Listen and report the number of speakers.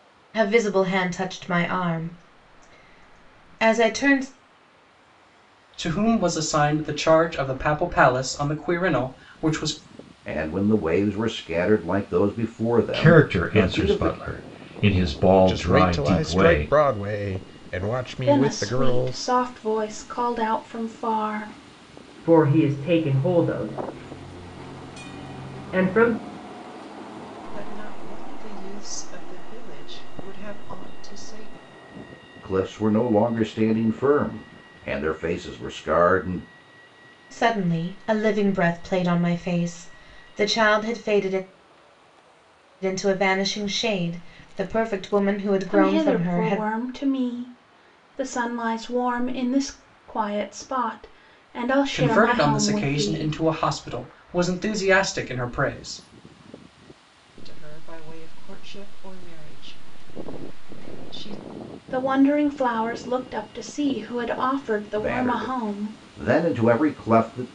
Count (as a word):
eight